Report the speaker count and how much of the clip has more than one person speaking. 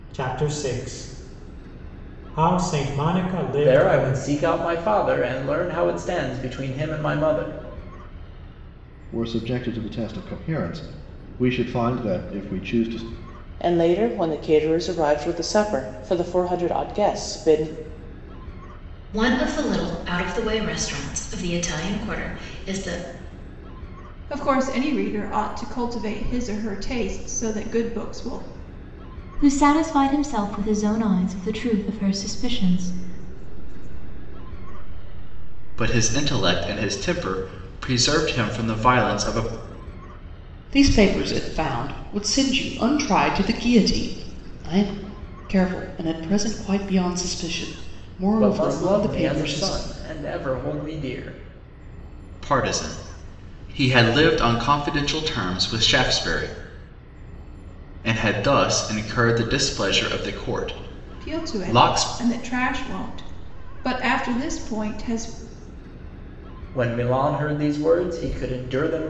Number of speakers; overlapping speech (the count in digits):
10, about 7%